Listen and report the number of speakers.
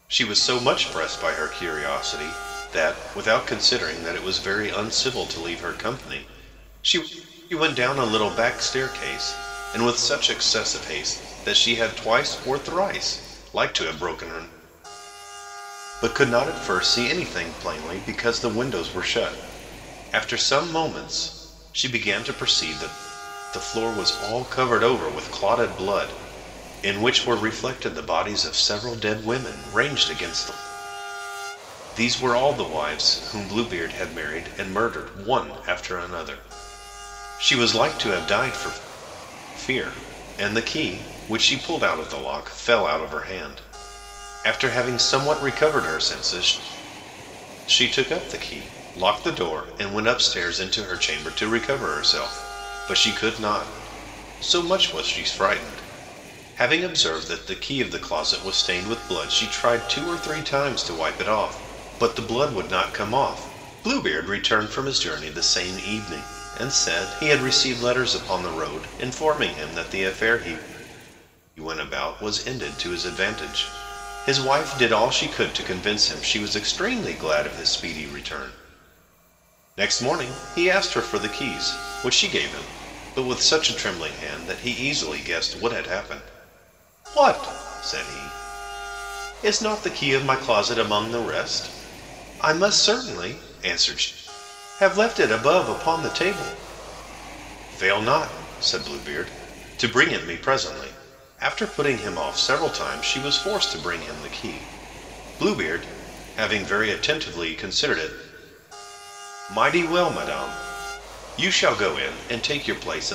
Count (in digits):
1